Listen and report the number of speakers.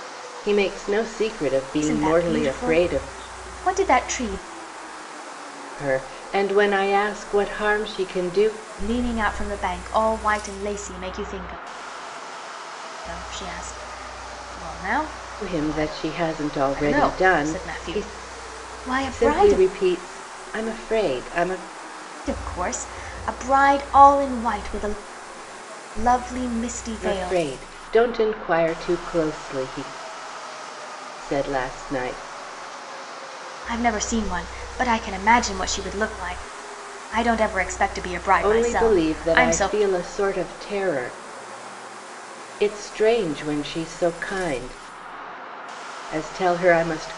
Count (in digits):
2